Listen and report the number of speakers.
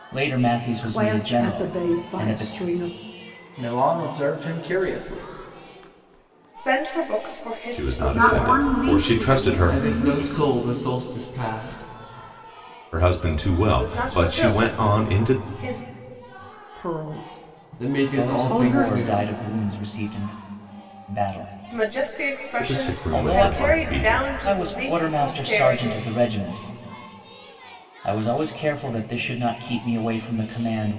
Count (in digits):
7